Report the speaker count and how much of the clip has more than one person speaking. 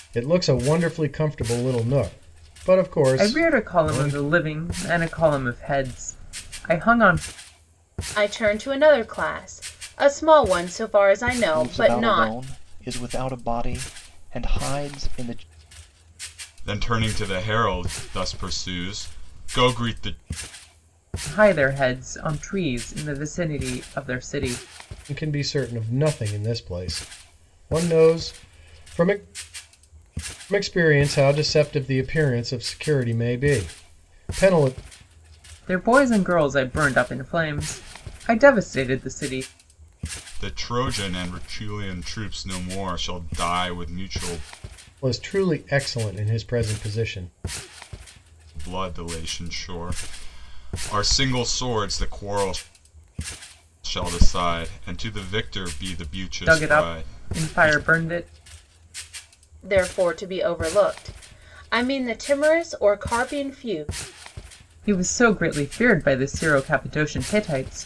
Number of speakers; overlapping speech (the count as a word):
five, about 5%